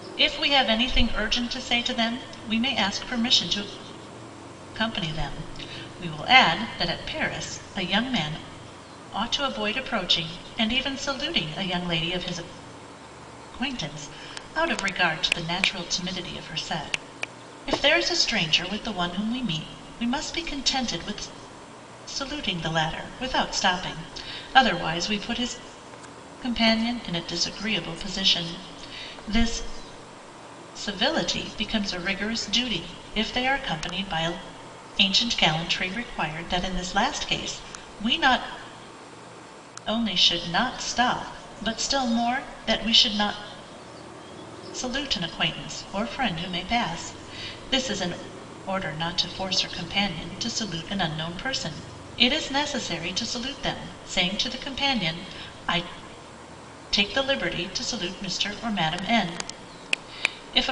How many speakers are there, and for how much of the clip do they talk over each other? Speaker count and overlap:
1, no overlap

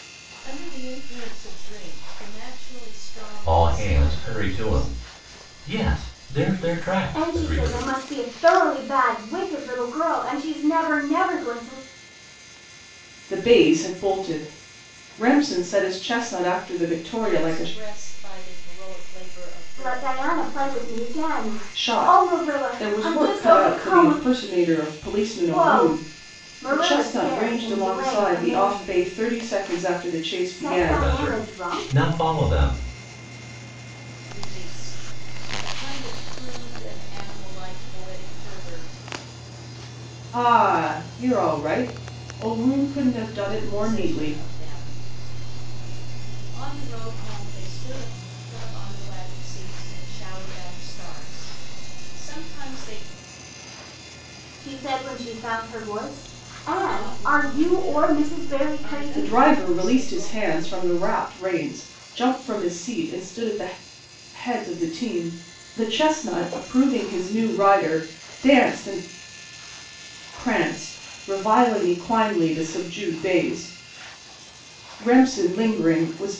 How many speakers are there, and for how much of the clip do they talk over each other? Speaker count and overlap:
4, about 22%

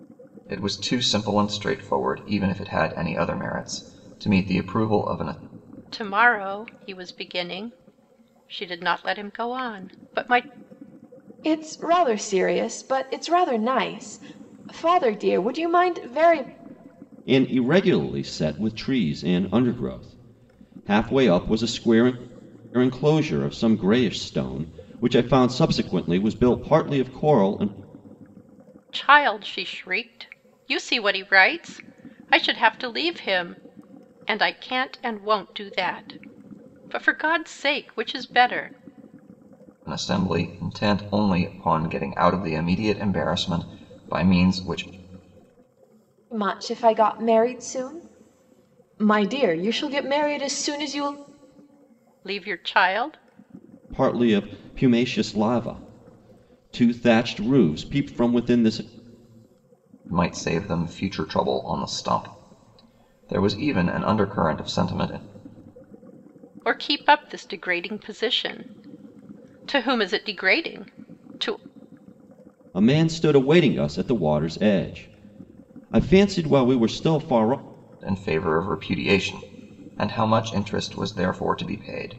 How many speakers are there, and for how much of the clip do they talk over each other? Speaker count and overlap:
4, no overlap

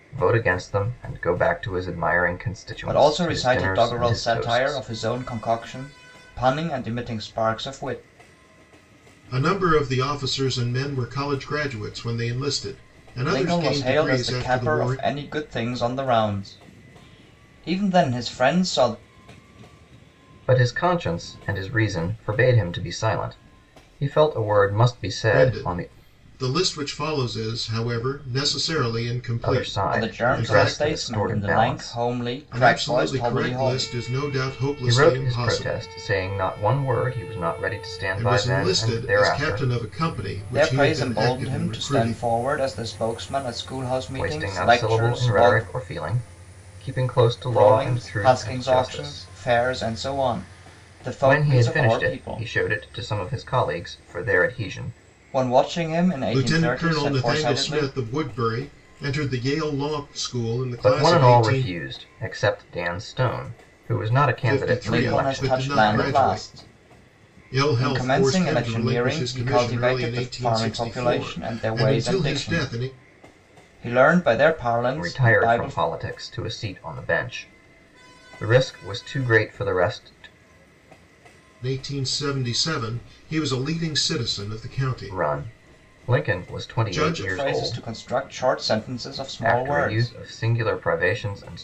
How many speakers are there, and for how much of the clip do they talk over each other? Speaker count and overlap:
3, about 35%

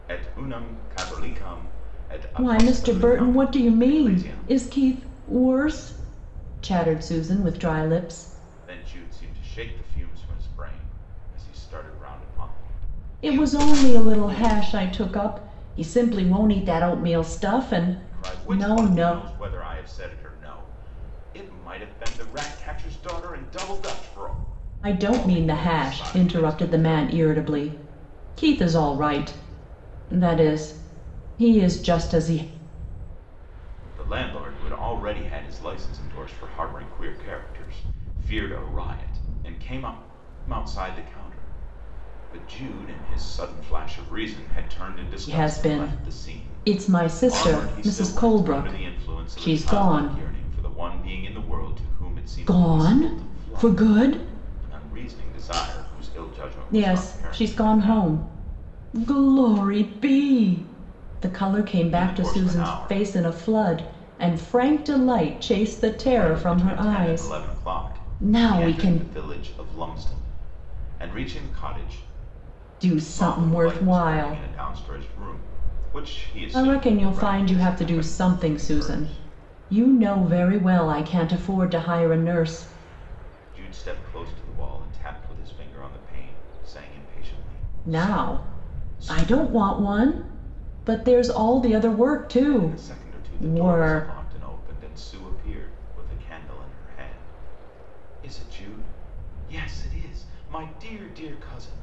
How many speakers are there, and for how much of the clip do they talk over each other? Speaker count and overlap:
2, about 25%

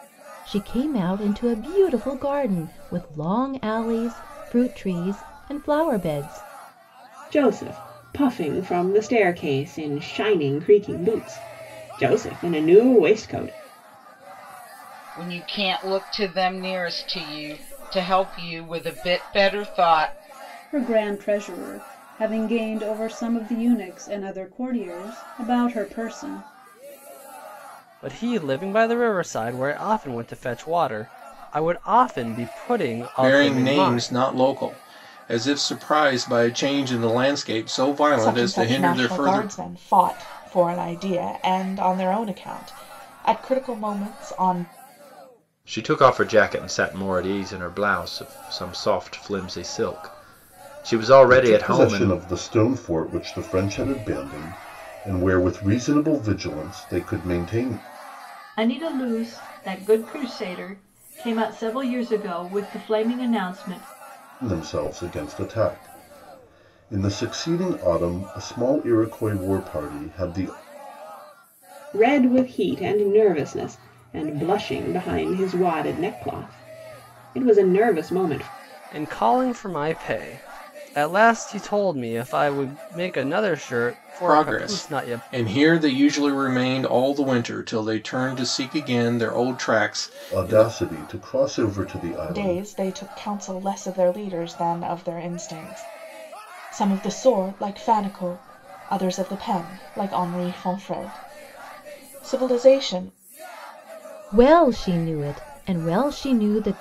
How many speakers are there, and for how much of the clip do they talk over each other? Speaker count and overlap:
10, about 5%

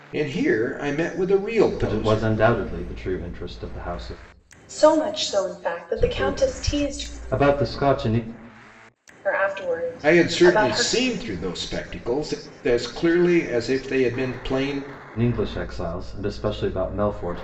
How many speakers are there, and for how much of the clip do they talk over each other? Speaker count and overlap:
3, about 15%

